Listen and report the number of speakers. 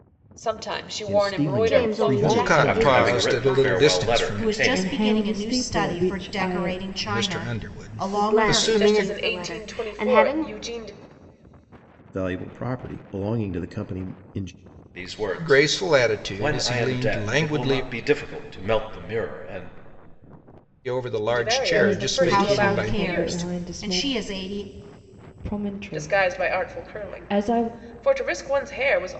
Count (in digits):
7